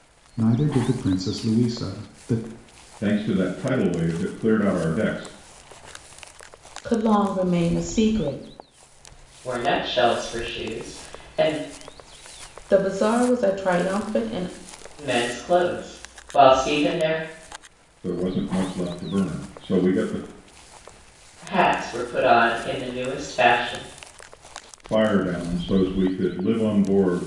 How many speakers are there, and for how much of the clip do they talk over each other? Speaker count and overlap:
4, no overlap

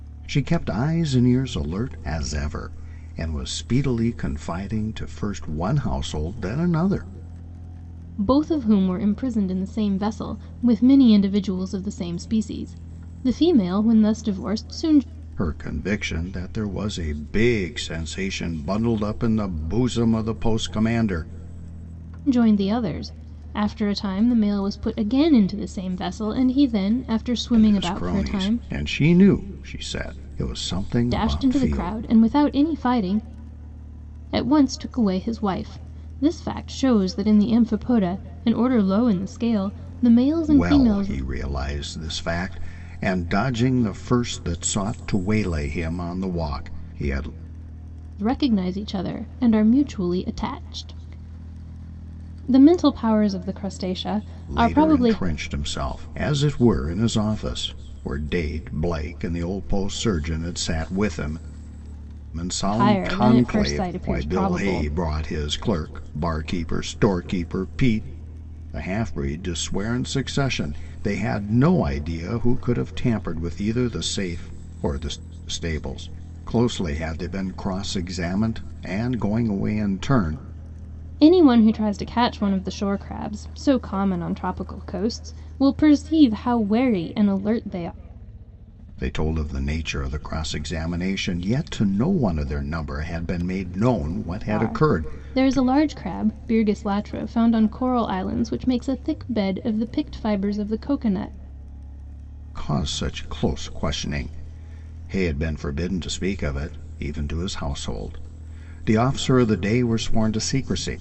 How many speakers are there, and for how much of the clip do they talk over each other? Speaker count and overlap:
2, about 6%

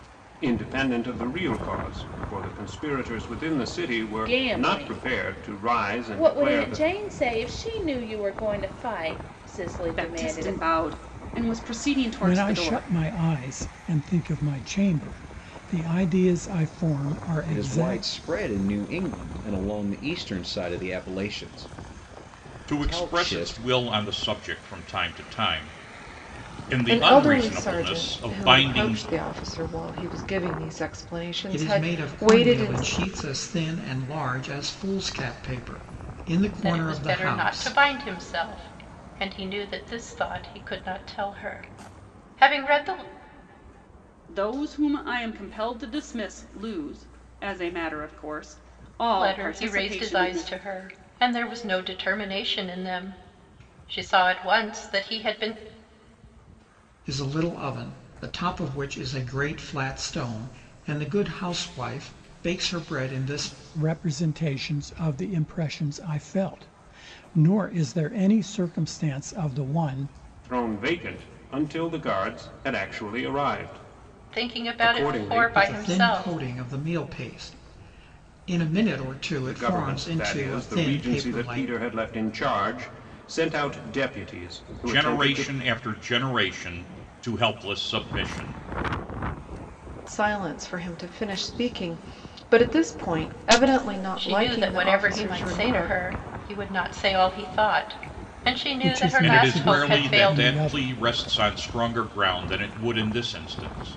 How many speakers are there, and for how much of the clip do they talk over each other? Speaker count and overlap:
9, about 21%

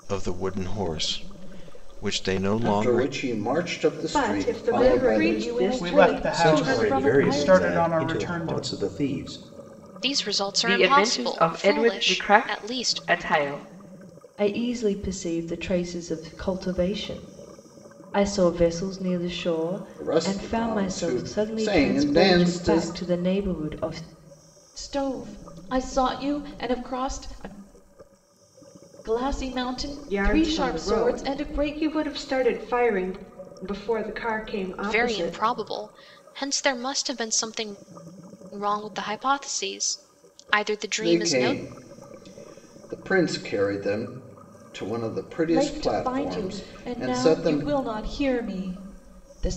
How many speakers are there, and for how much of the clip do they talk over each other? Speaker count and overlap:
9, about 32%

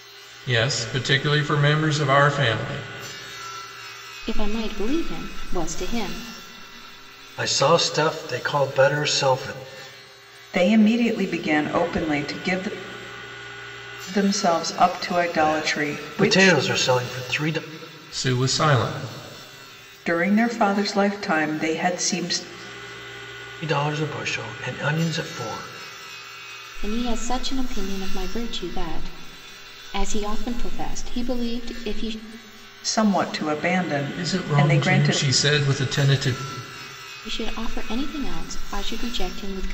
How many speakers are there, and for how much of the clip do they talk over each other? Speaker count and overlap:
4, about 6%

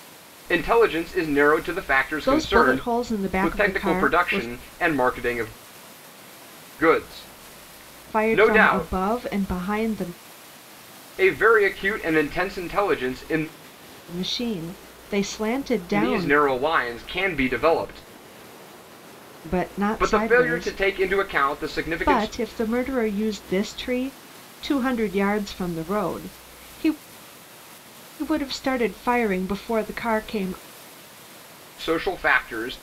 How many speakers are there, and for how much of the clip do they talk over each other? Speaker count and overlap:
2, about 13%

